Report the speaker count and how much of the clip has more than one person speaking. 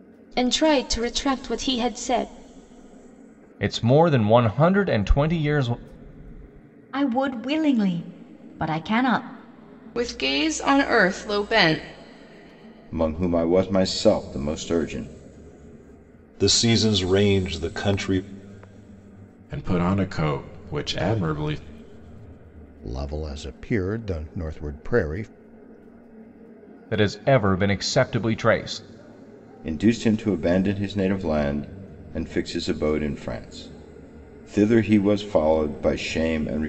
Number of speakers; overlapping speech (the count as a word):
eight, no overlap